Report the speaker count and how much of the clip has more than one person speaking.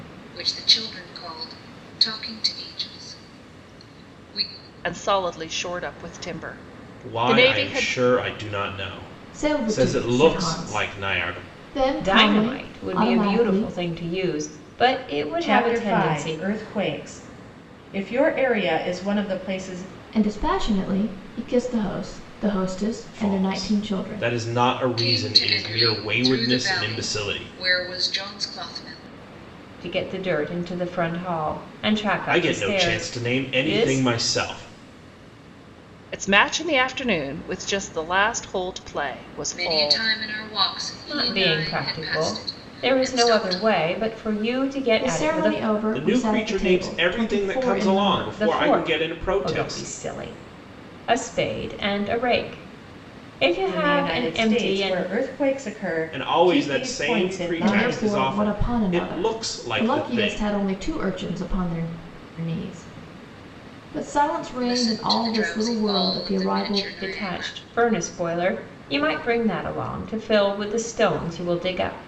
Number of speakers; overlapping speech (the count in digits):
6, about 39%